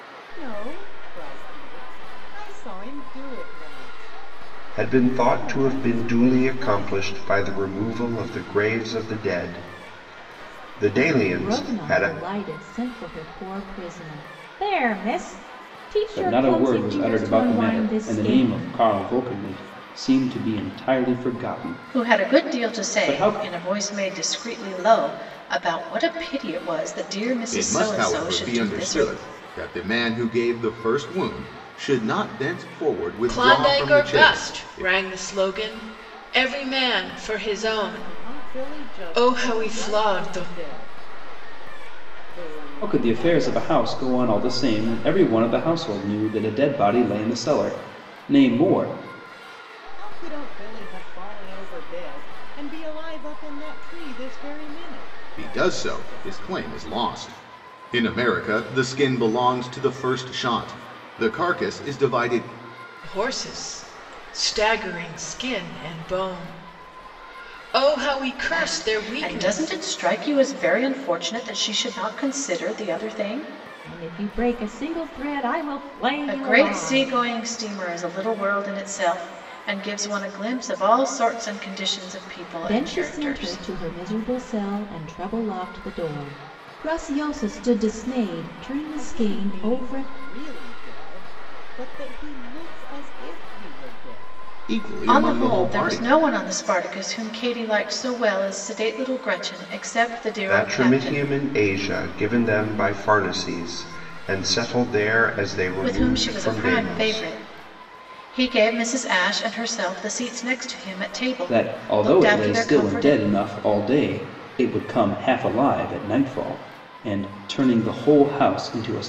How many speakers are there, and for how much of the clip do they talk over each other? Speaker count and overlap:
seven, about 23%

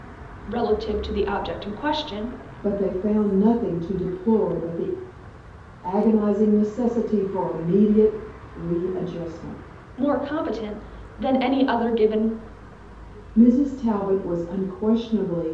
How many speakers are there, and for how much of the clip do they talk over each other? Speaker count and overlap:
two, no overlap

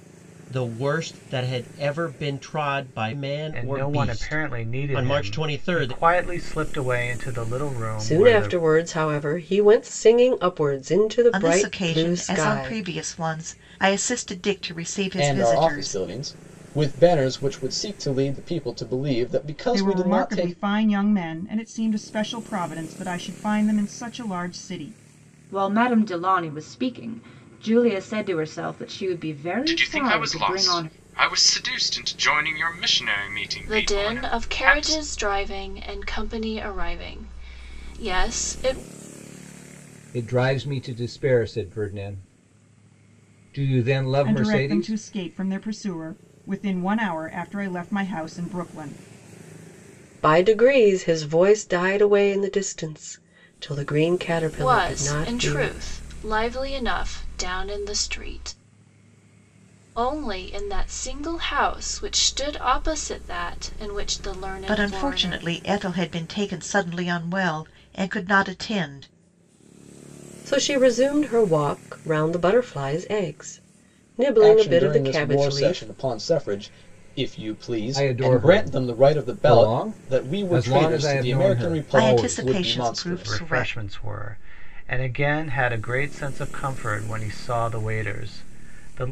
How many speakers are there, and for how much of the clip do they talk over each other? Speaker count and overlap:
ten, about 21%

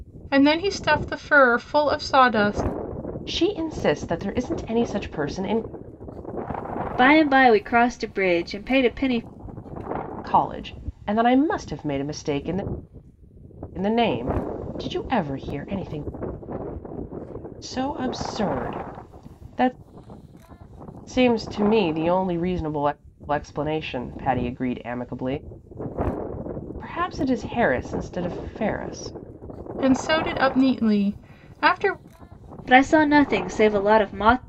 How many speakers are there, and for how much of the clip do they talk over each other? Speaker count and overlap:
three, no overlap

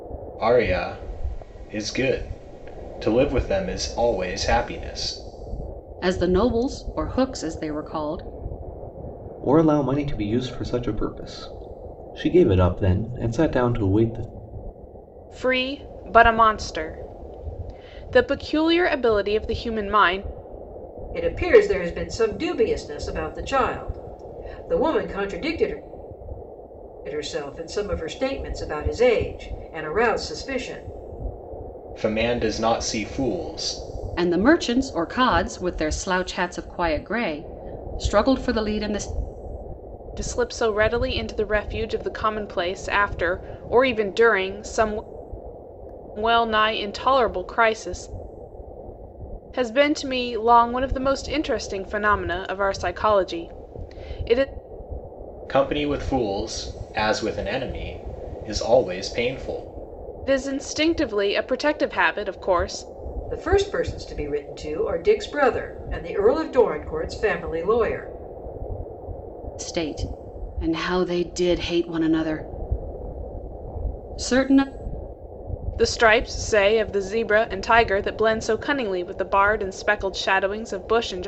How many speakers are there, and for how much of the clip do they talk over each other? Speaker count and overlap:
five, no overlap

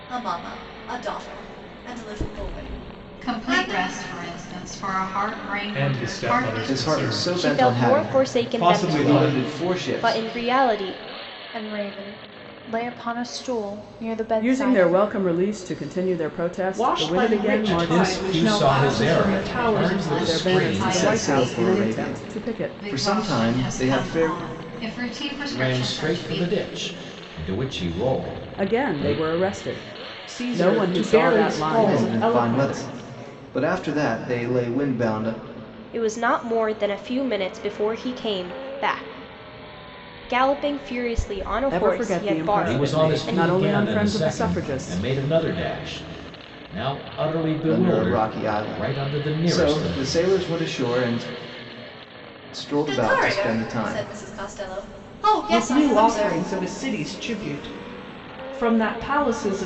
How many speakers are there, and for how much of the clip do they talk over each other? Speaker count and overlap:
nine, about 43%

